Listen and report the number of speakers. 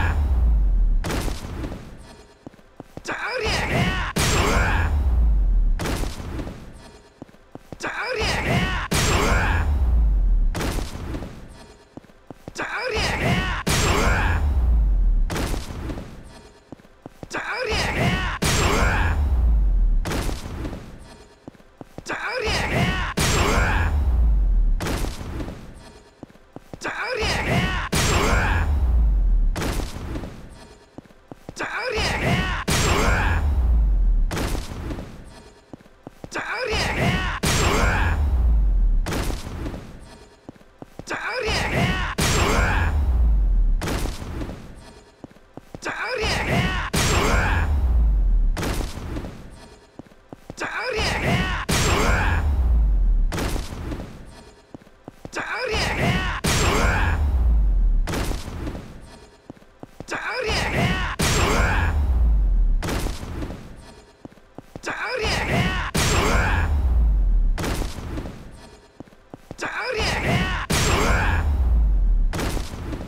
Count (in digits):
0